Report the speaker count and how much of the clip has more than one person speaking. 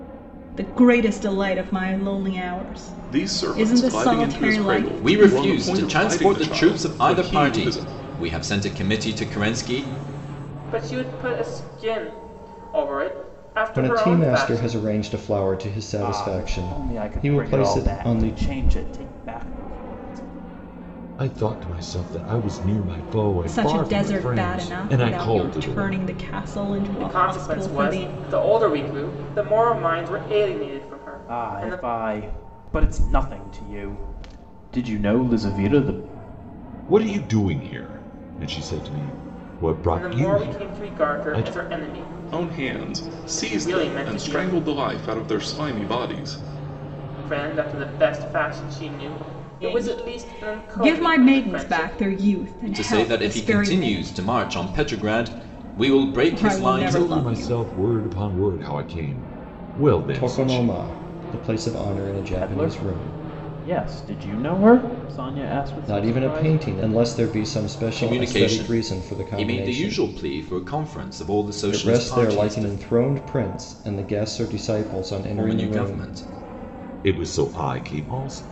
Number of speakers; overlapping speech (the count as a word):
seven, about 36%